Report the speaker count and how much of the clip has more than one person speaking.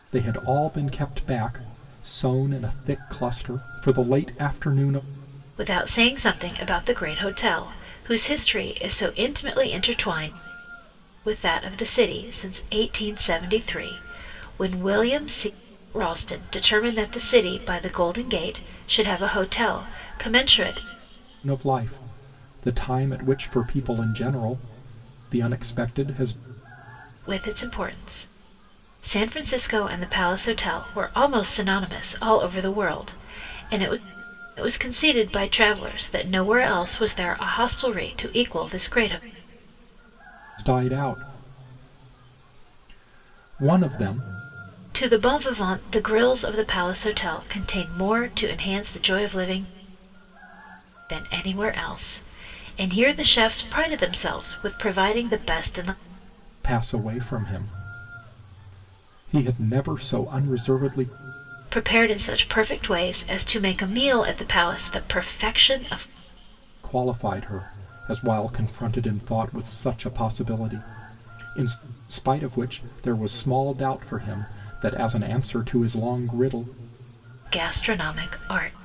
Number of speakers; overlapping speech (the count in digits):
2, no overlap